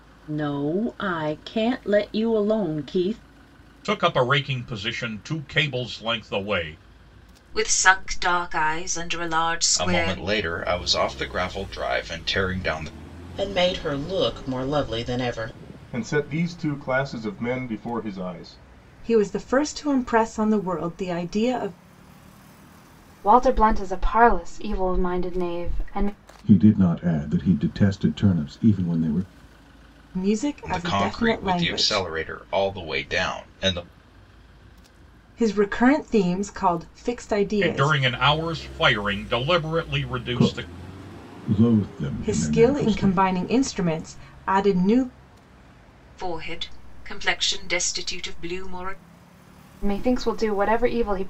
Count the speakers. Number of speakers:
9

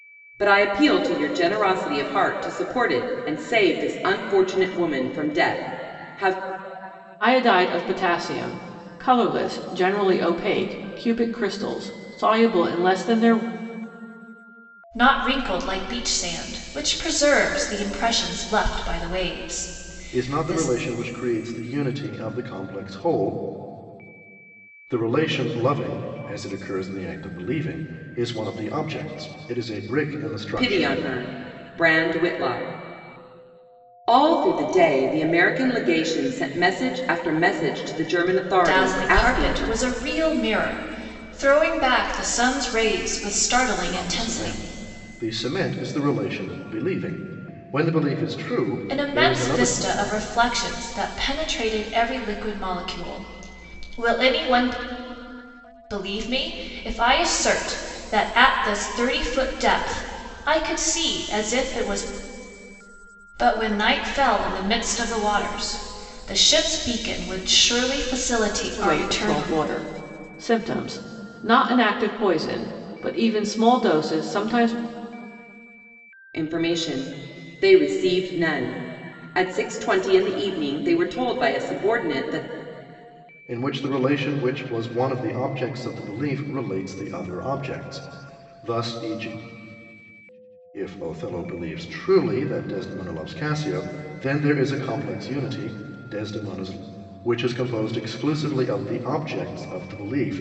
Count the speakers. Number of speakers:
4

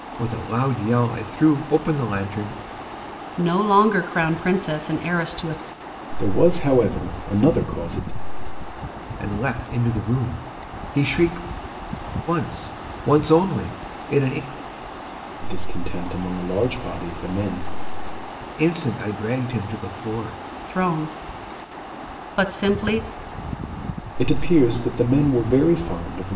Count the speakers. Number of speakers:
3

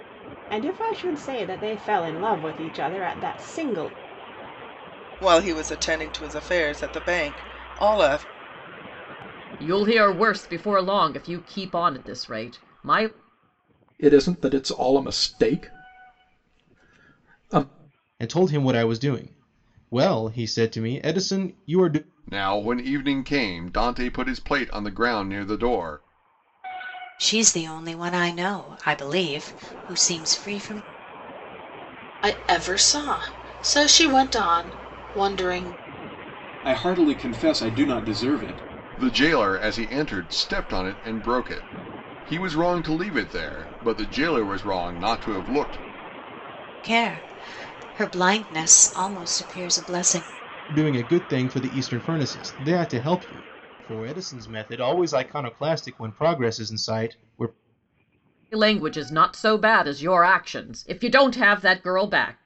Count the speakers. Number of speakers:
9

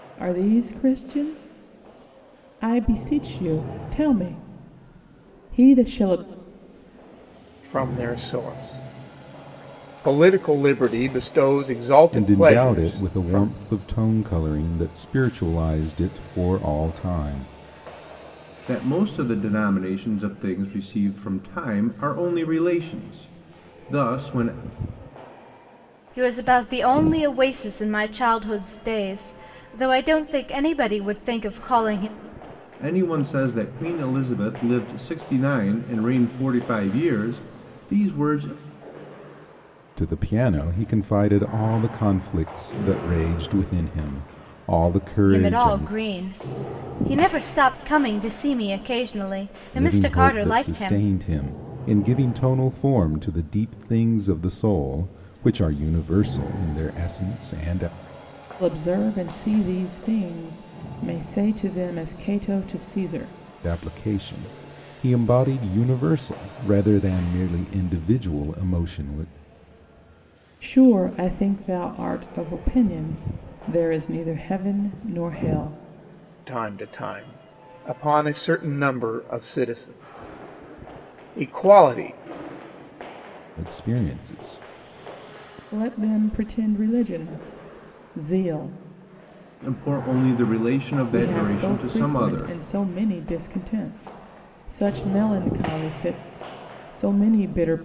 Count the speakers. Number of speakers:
5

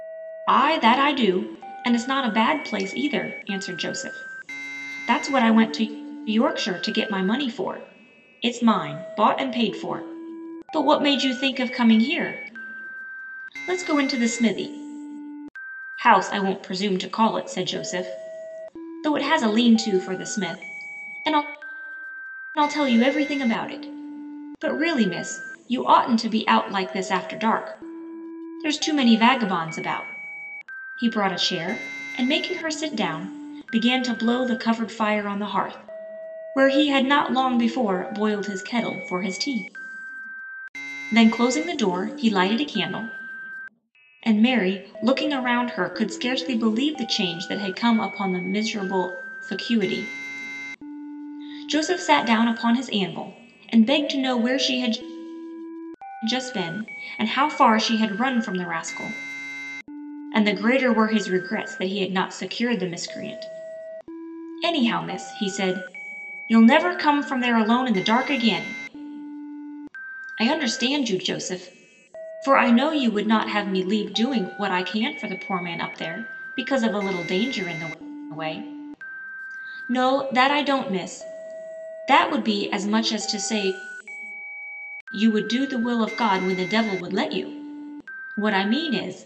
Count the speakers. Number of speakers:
1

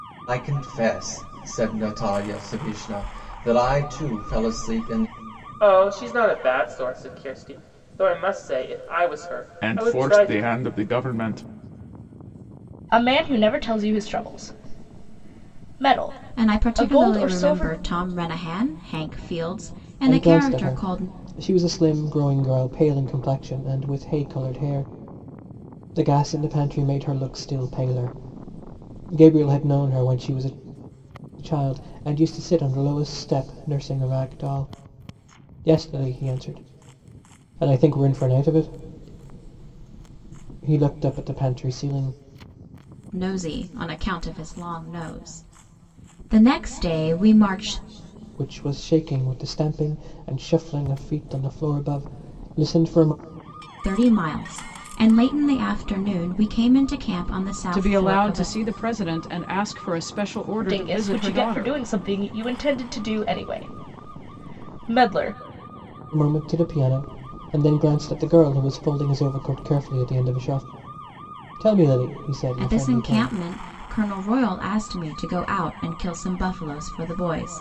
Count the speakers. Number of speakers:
6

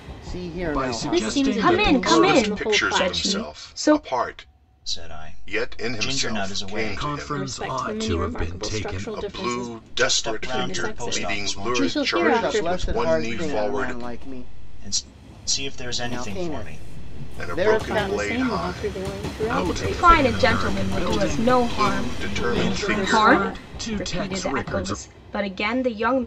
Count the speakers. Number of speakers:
6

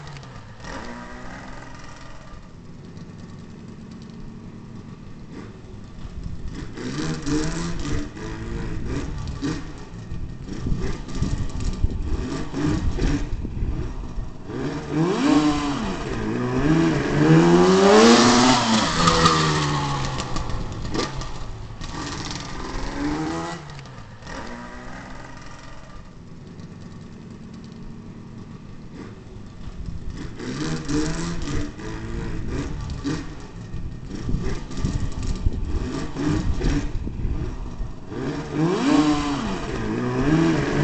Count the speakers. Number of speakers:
0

